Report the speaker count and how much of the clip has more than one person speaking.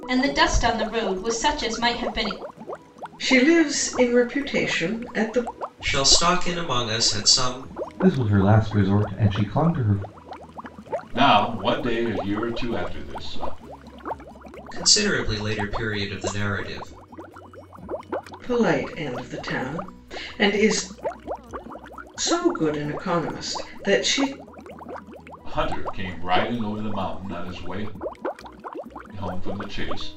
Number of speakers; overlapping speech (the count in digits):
5, no overlap